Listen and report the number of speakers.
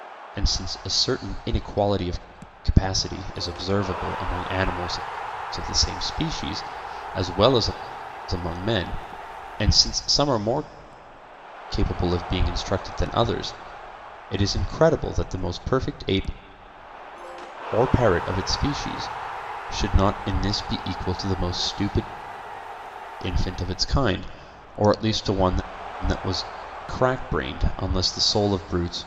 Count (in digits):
1